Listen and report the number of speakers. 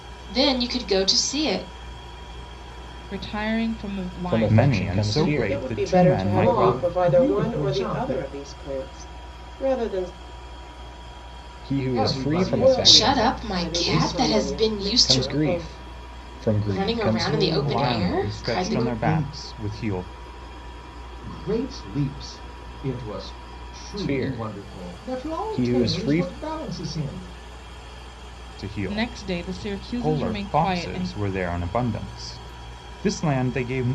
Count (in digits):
6